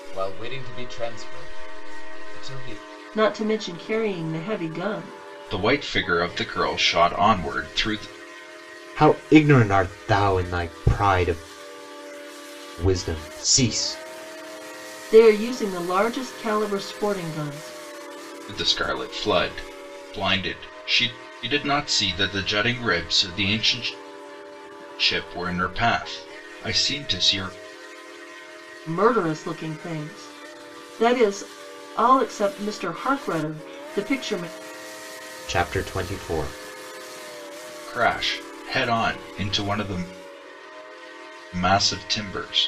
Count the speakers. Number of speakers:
4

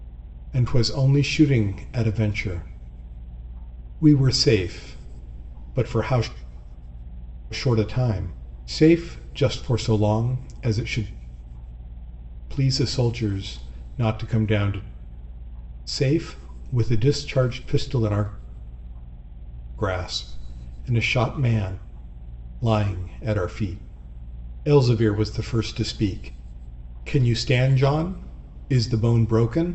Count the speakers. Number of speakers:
1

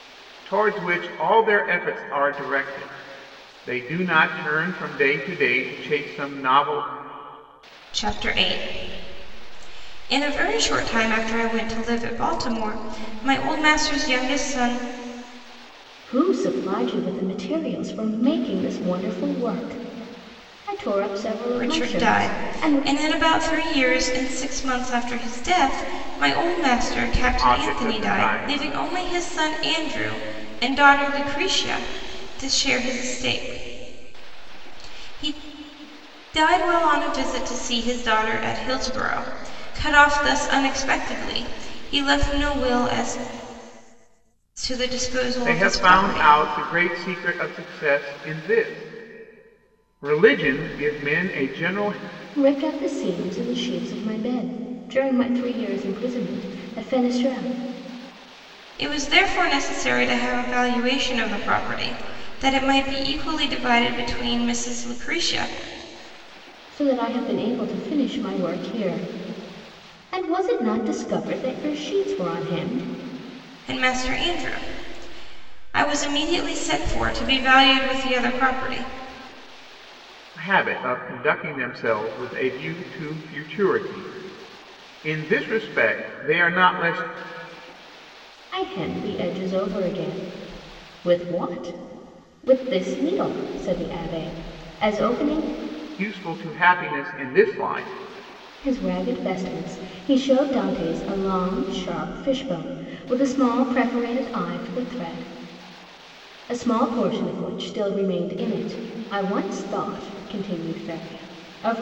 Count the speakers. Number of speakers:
3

